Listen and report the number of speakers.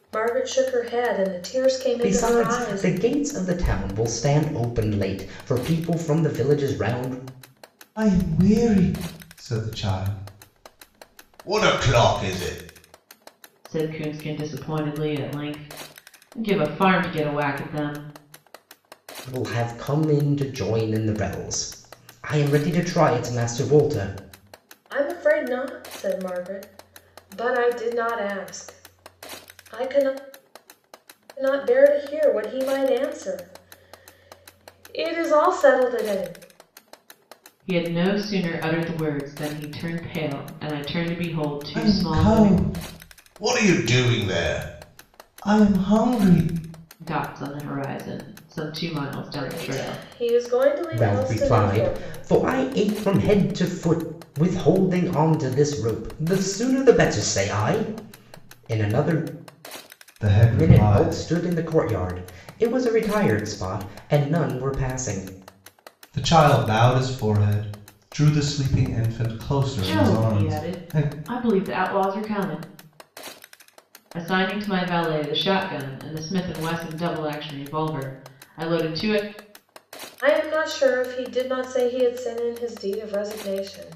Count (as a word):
four